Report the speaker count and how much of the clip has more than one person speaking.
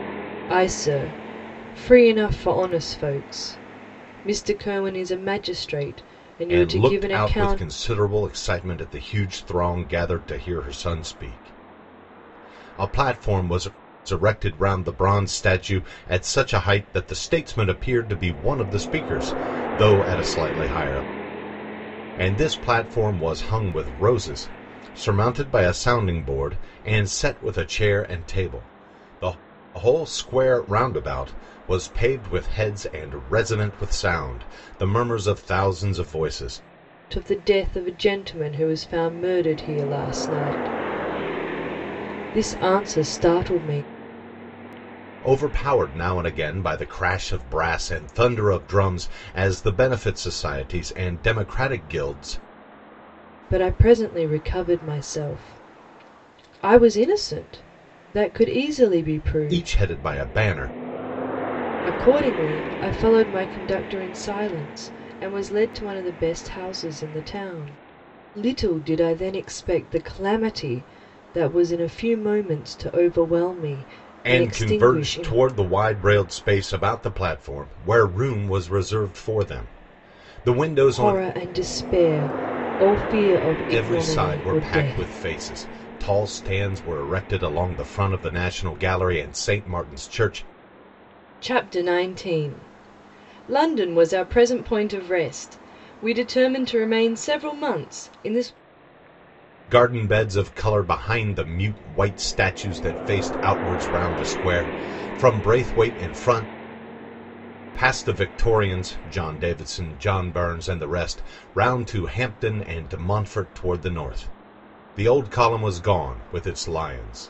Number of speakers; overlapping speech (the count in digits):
2, about 4%